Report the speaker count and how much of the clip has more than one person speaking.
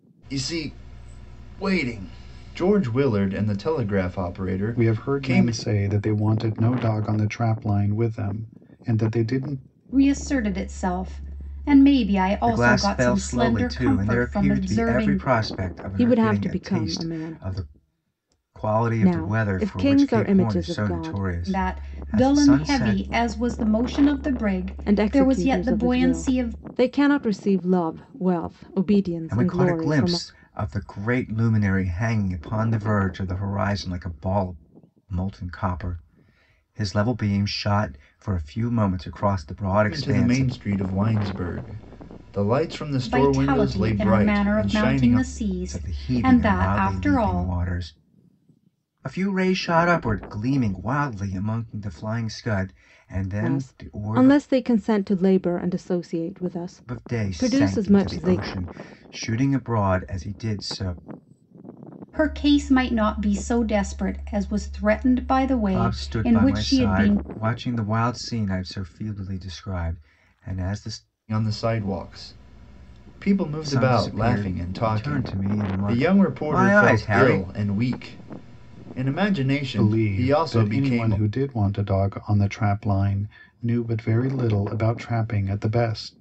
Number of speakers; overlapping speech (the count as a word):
five, about 30%